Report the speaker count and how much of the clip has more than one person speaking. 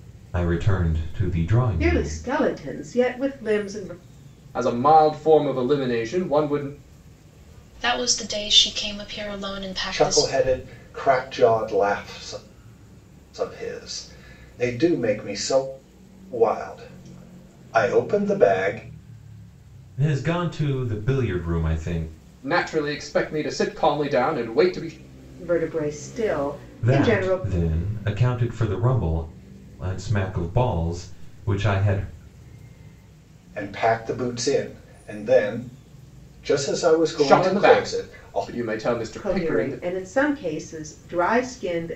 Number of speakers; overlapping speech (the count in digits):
5, about 8%